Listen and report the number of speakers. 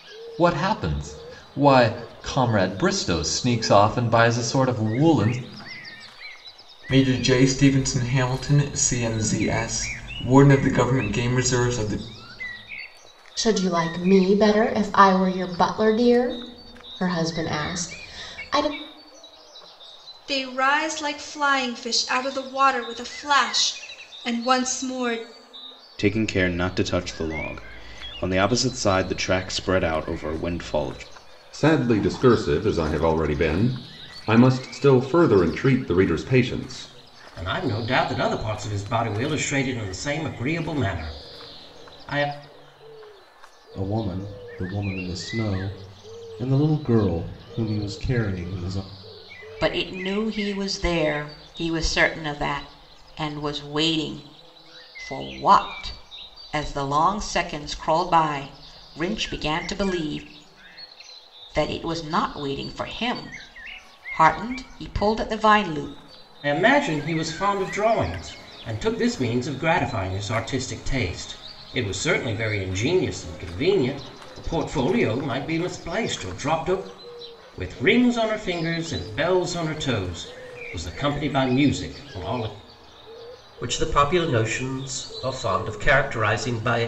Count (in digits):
9